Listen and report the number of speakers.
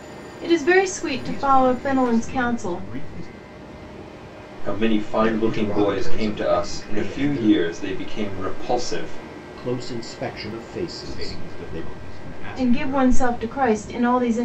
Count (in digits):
4